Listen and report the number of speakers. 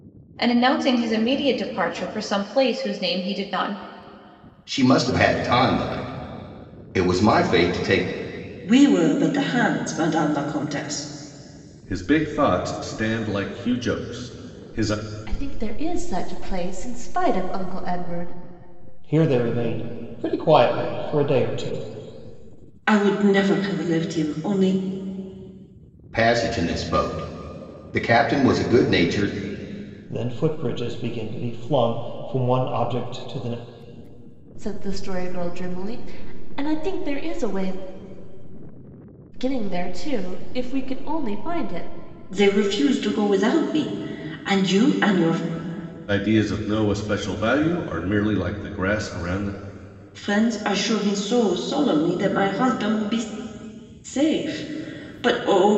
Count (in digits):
6